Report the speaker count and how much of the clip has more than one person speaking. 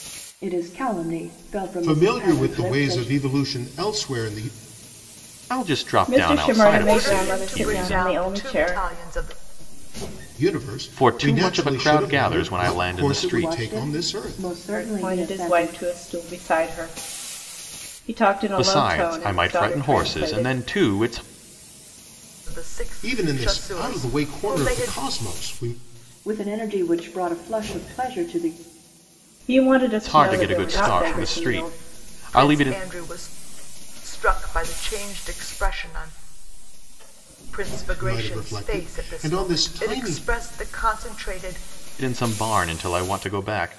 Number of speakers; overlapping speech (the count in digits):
5, about 41%